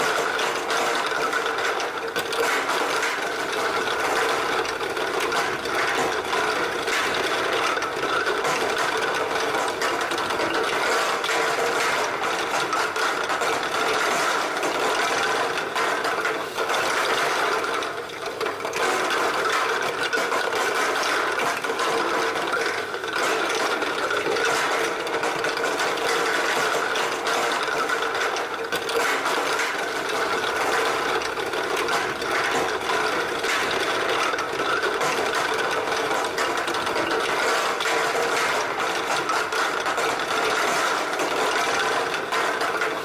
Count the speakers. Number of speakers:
zero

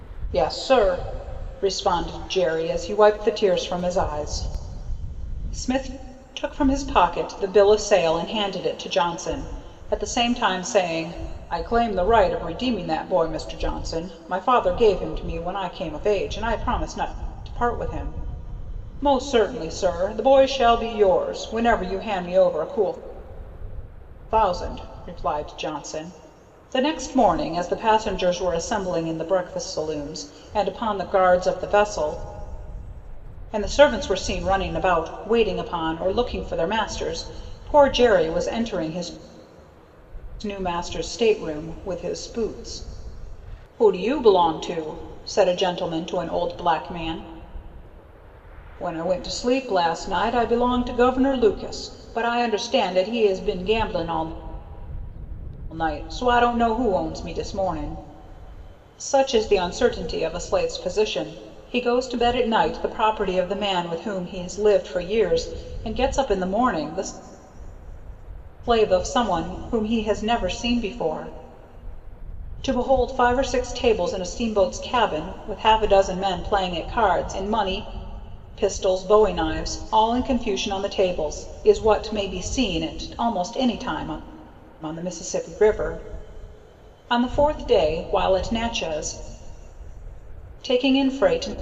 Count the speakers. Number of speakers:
one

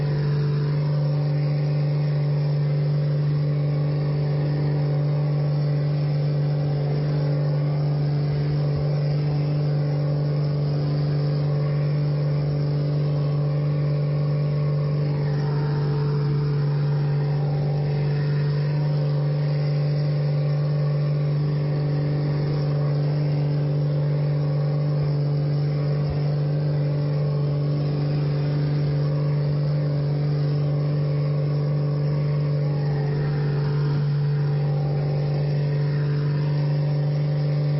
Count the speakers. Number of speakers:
zero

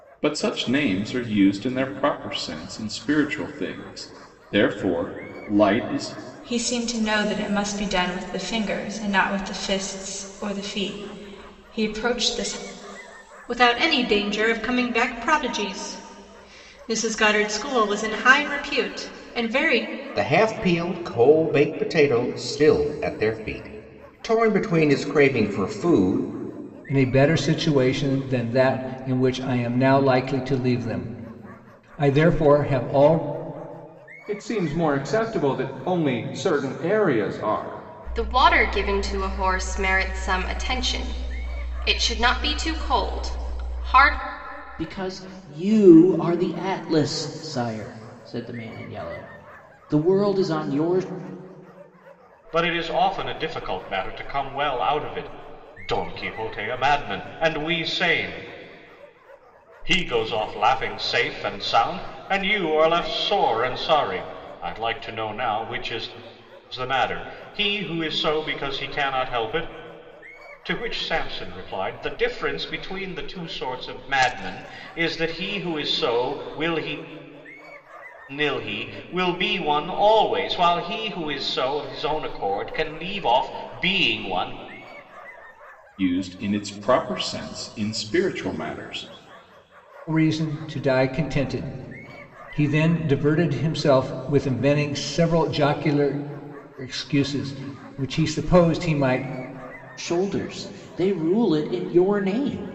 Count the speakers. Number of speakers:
nine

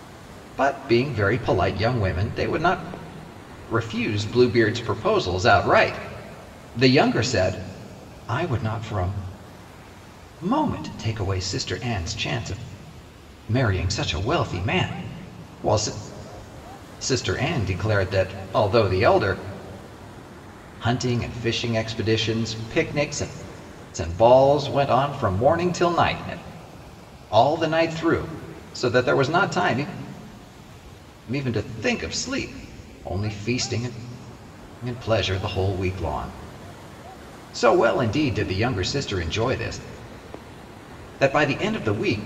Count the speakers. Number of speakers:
one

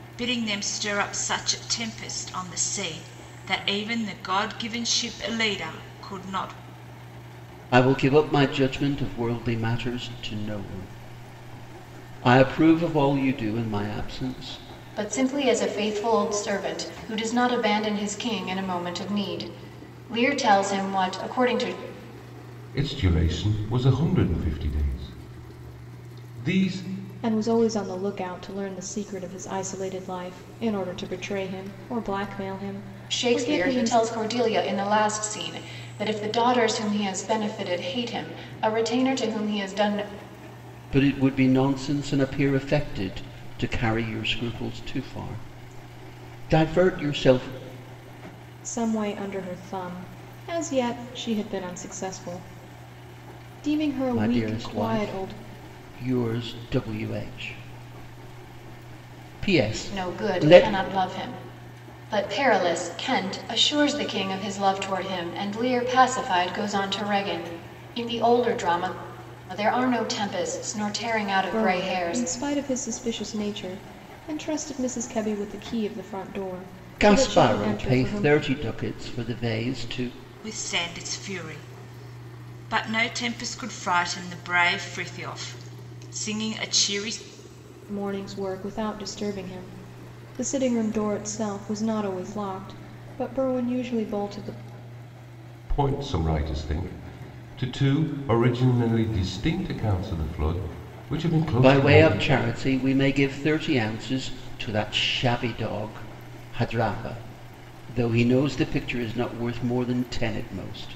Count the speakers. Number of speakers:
five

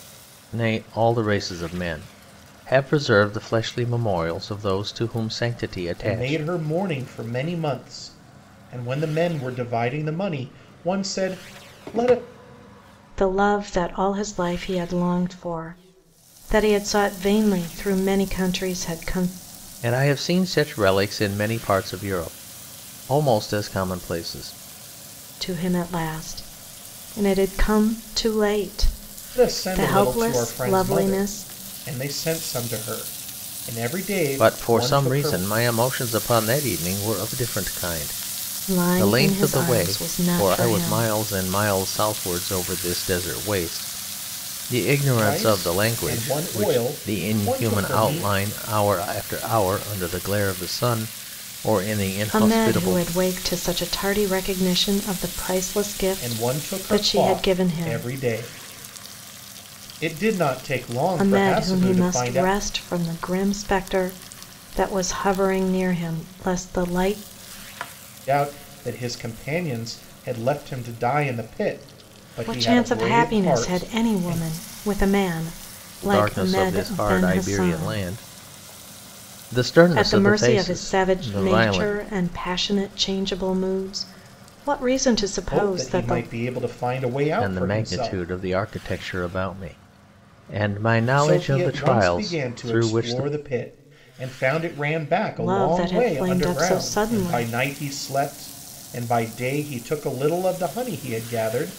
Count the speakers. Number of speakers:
three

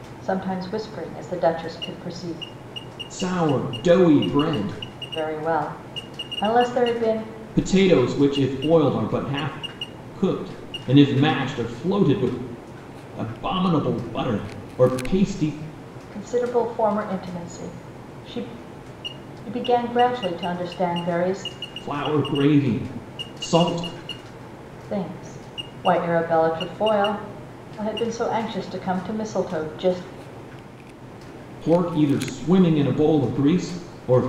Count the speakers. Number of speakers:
two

